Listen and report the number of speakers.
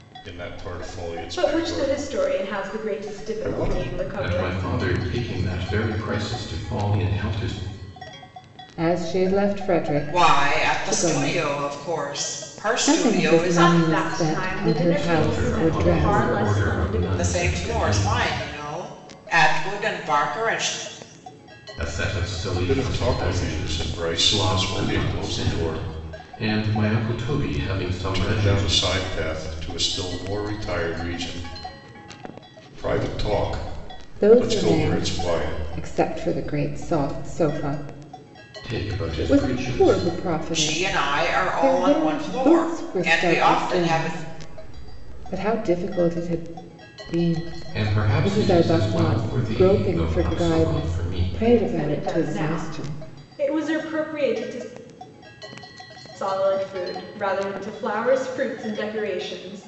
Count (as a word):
five